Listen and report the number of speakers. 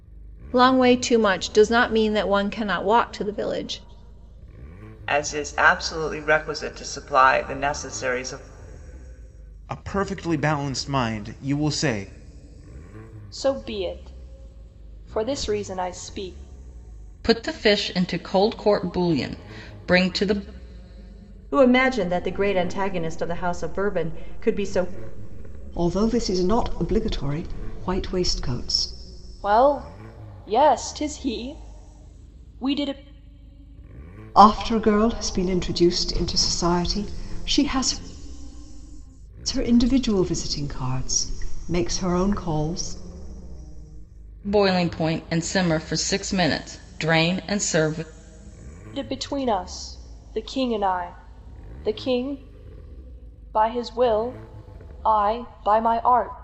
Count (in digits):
7